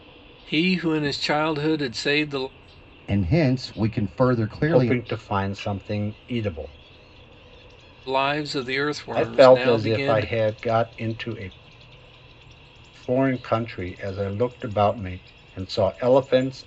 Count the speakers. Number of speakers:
three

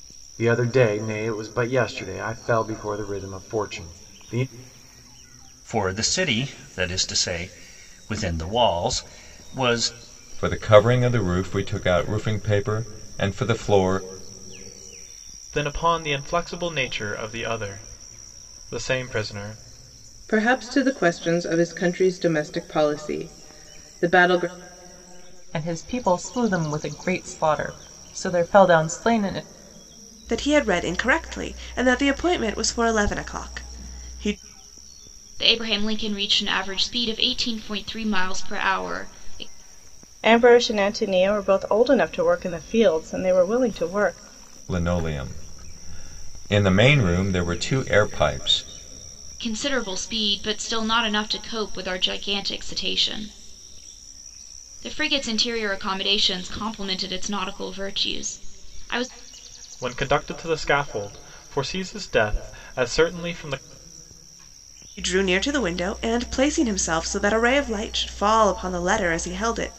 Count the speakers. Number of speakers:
nine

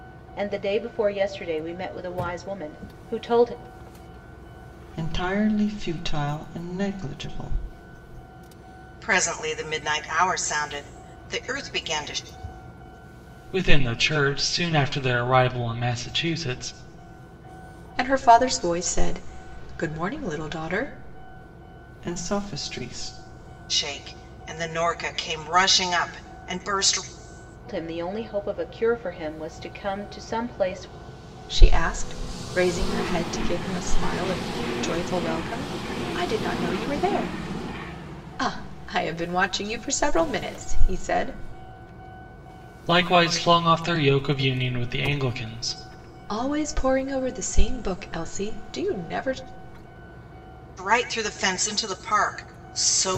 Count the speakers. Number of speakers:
five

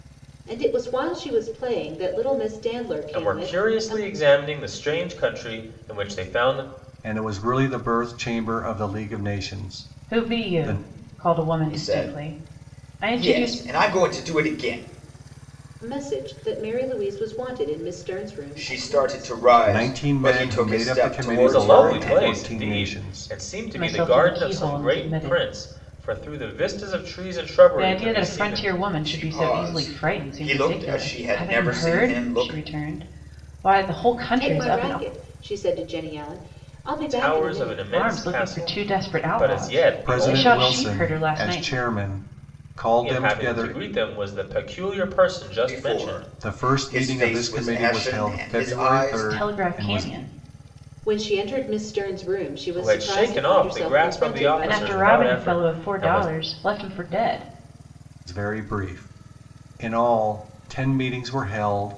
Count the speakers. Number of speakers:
five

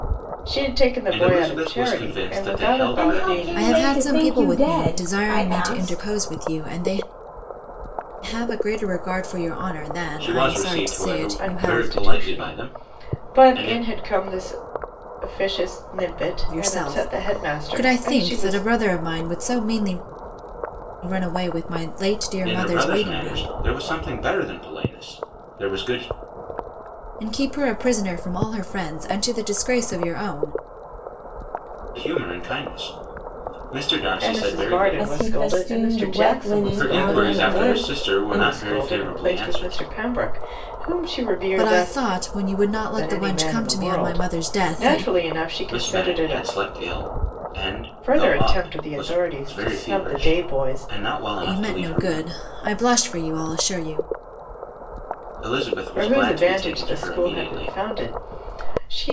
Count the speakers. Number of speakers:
four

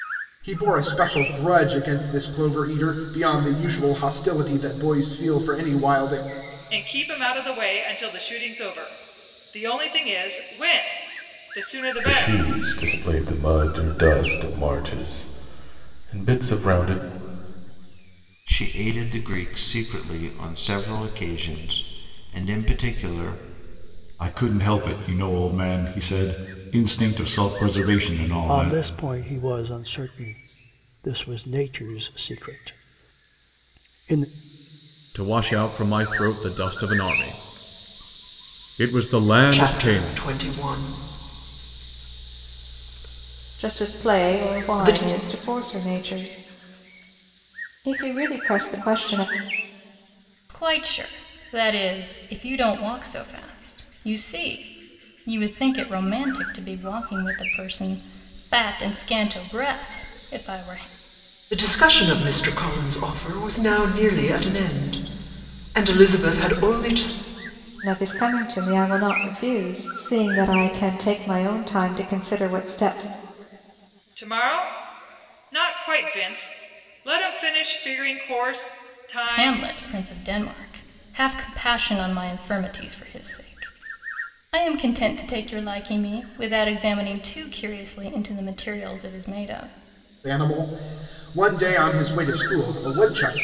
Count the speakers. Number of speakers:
ten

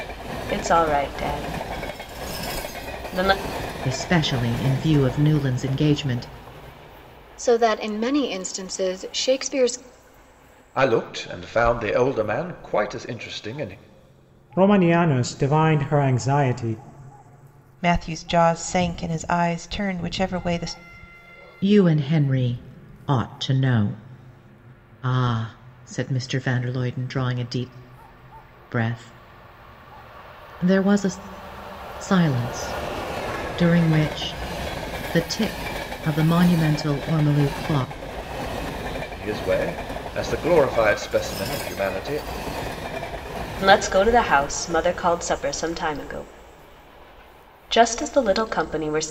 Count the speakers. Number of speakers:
six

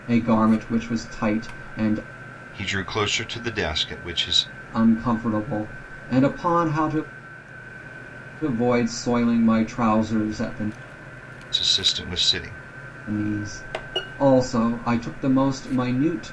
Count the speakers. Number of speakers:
two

